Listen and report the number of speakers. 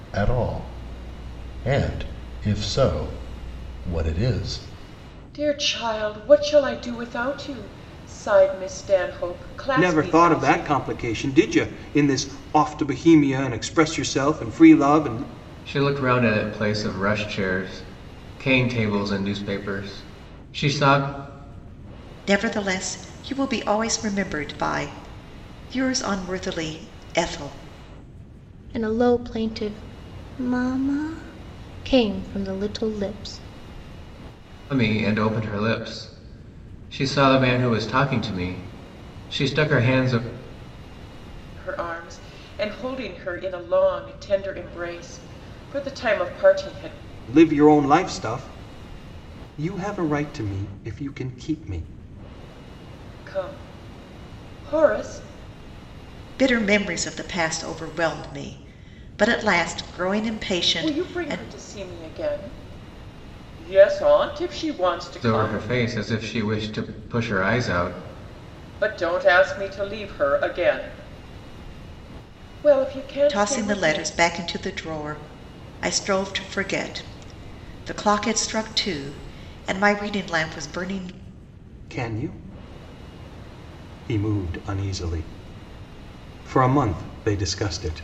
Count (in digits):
6